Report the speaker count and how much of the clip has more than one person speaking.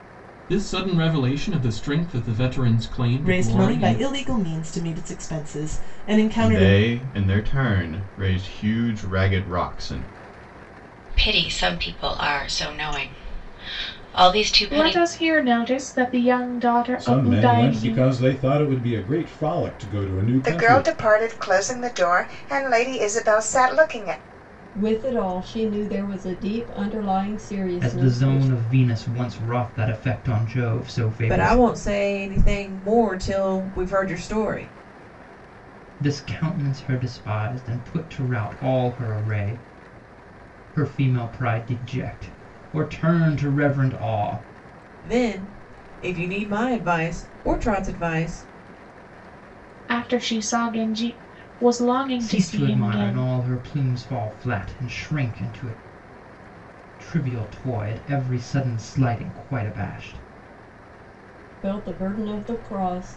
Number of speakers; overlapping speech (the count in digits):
10, about 9%